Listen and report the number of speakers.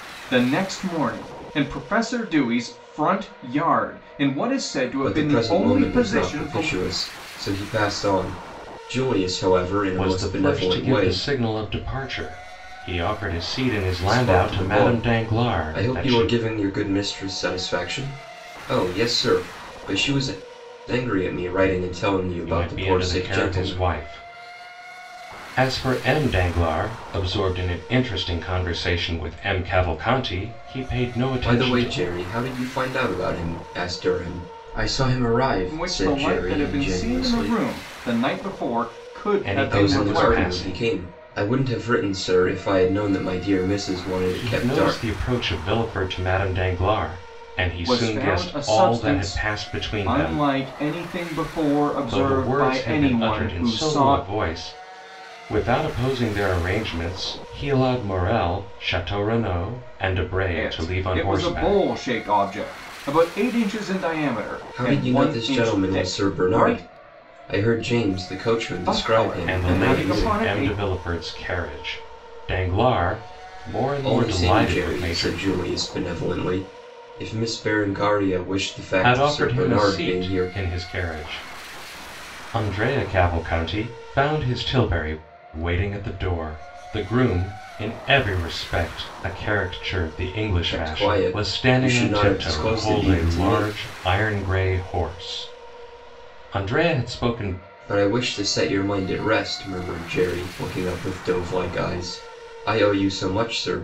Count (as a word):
three